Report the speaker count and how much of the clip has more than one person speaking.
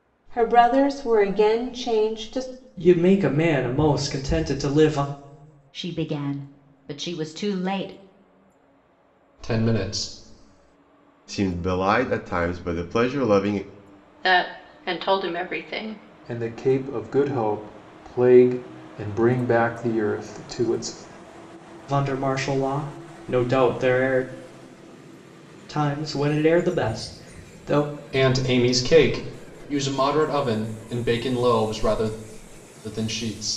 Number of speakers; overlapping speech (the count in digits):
7, no overlap